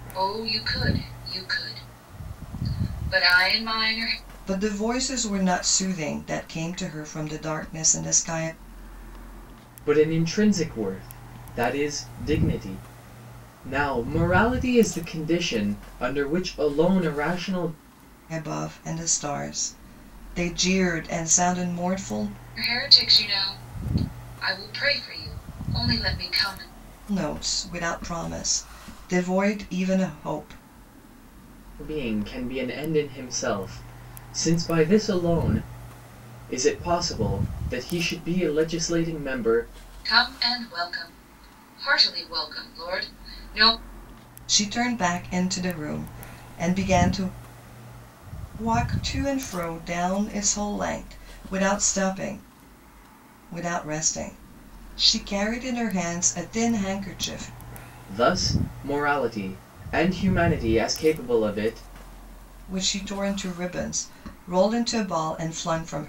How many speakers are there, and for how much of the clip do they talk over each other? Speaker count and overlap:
3, no overlap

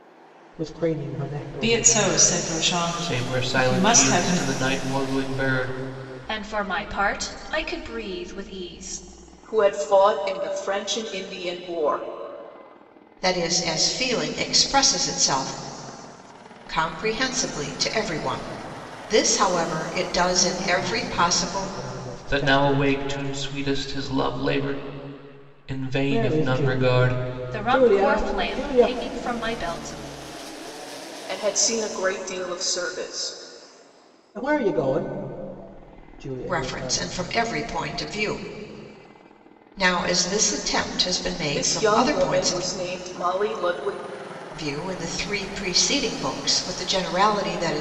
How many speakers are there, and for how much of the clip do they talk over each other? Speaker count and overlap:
6, about 19%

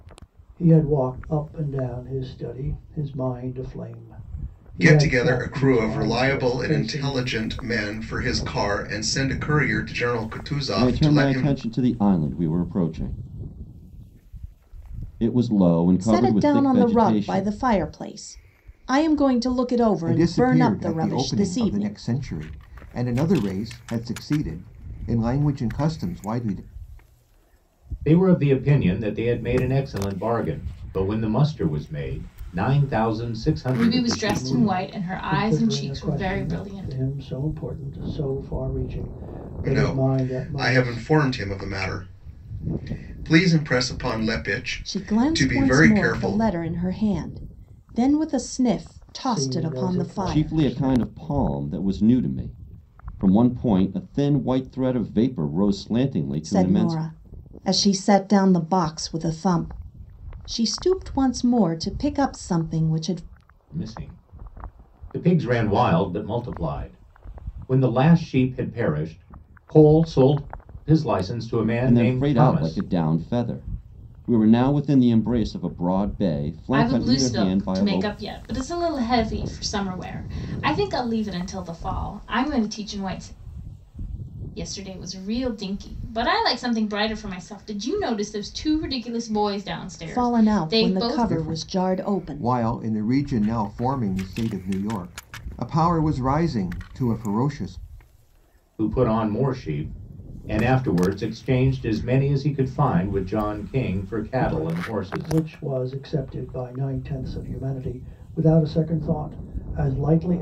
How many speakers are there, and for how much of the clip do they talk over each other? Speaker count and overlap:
7, about 20%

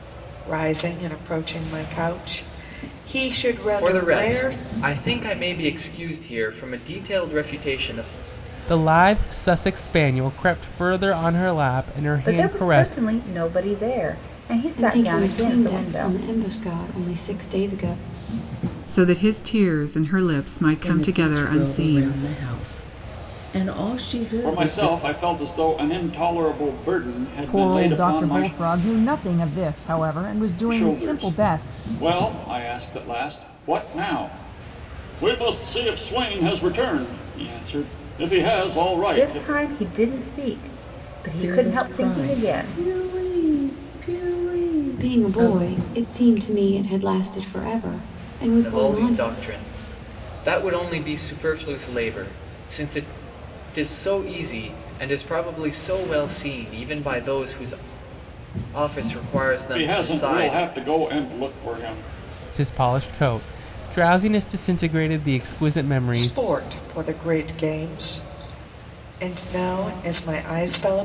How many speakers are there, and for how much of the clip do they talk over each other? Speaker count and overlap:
9, about 17%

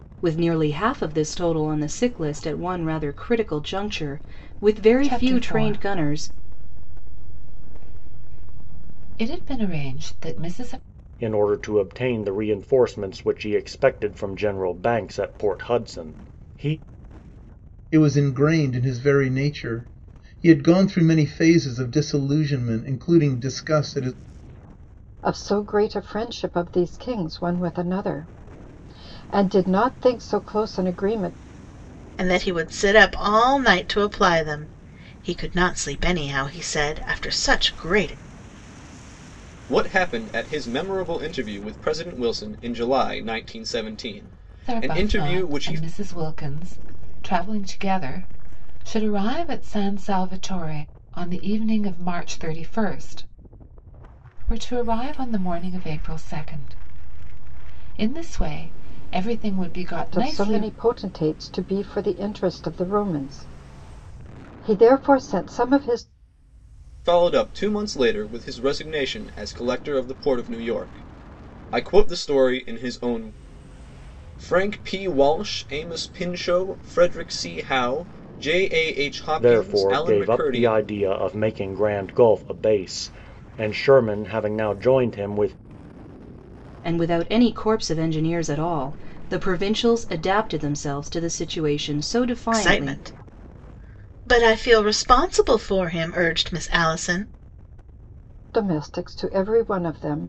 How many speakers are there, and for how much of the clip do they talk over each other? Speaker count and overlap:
7, about 5%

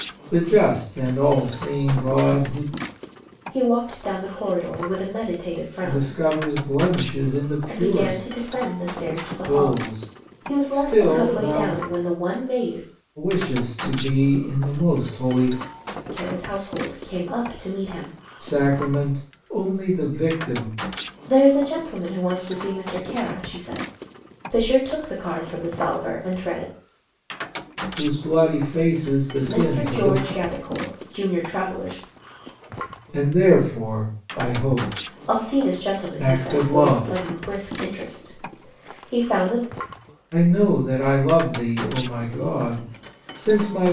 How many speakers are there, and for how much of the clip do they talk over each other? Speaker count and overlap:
2, about 12%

